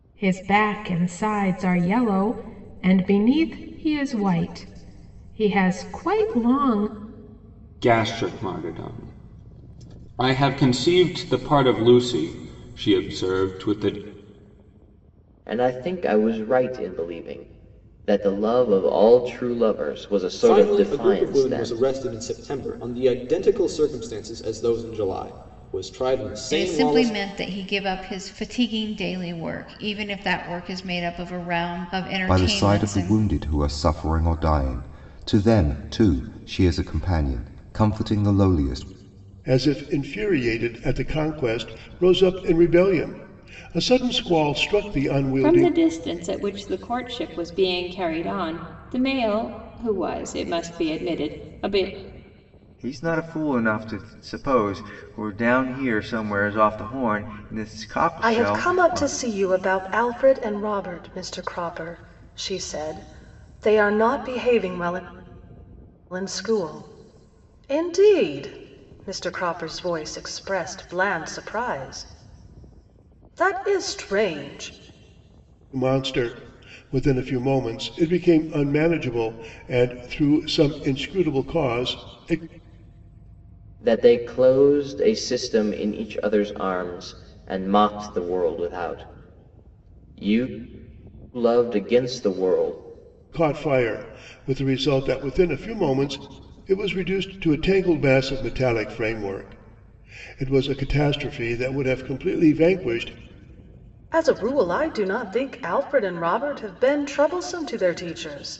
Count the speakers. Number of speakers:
10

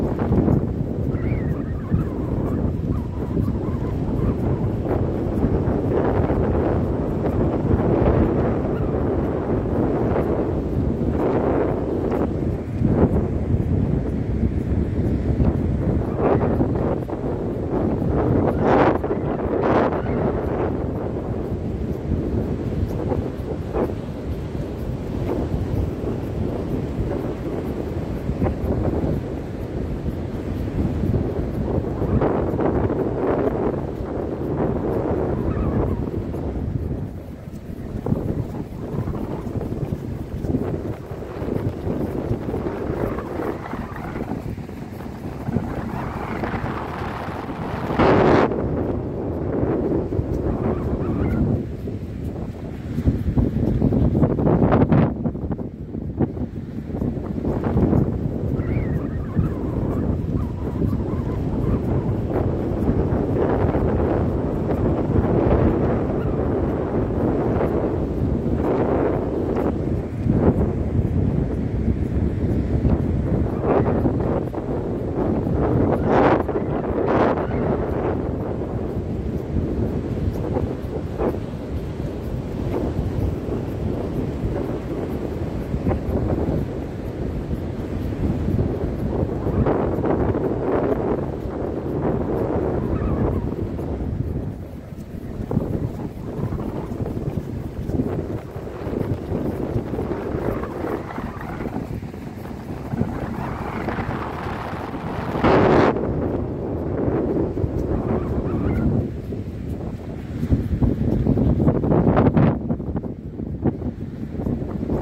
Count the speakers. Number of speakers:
0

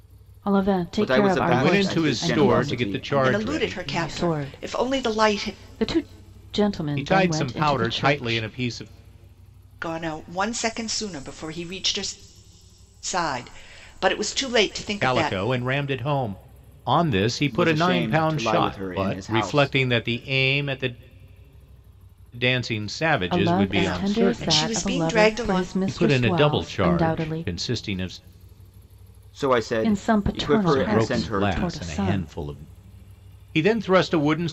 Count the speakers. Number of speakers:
4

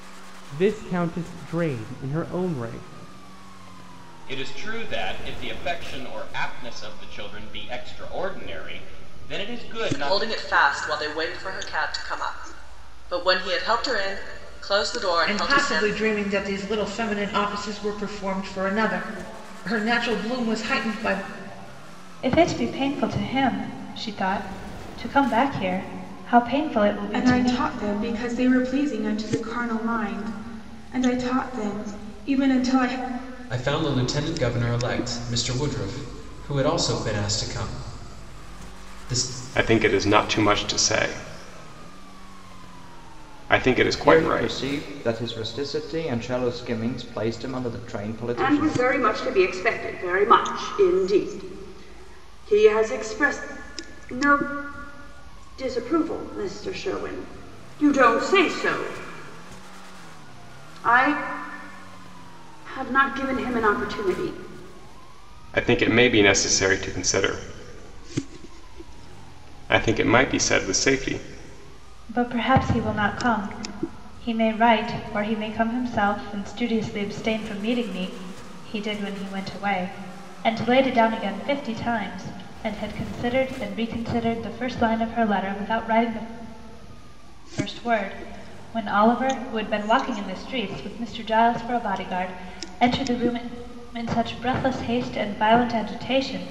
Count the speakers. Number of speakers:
10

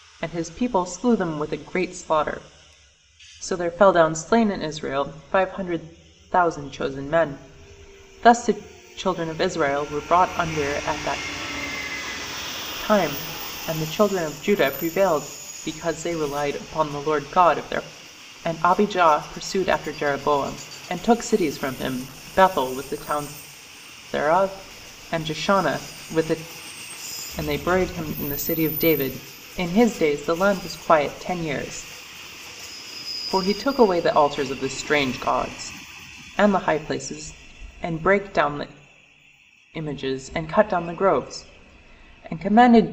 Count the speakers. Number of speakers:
1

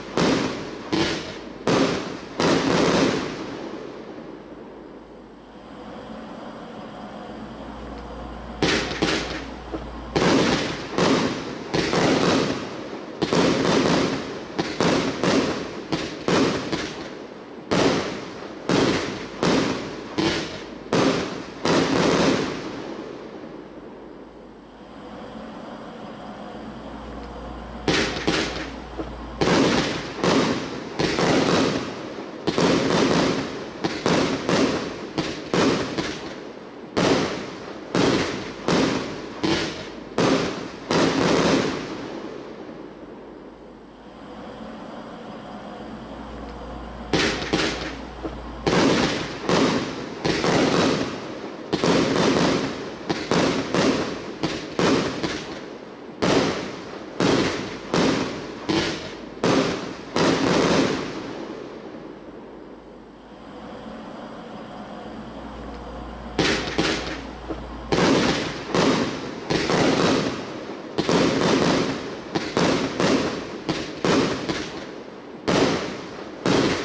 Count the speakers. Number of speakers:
0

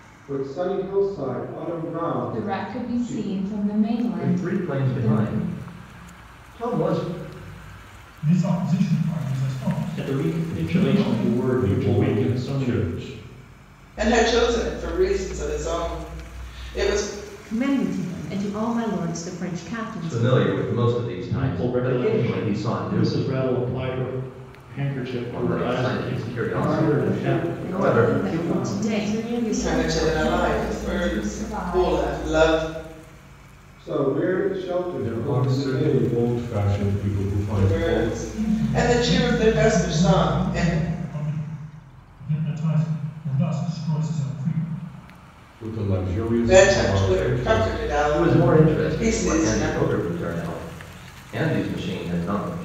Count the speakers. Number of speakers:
8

